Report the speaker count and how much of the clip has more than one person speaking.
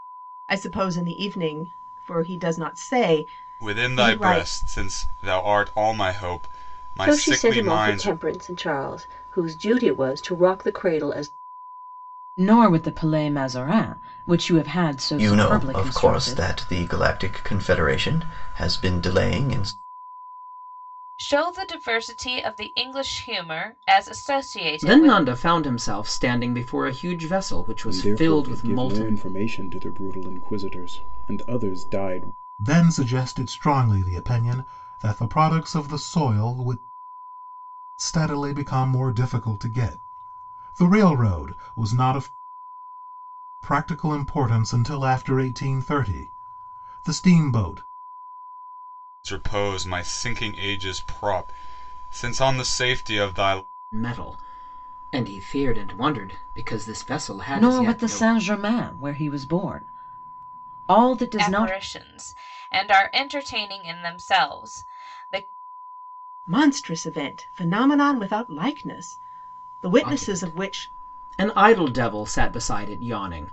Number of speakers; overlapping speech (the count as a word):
nine, about 10%